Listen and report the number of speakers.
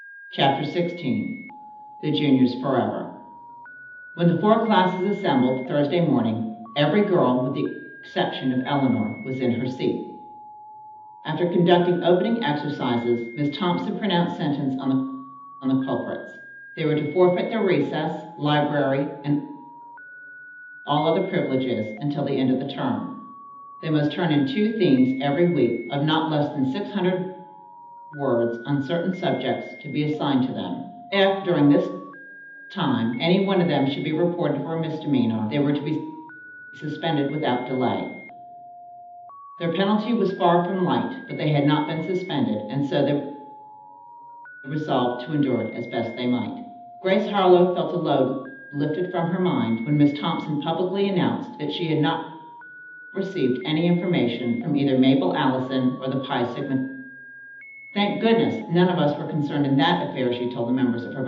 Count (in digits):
1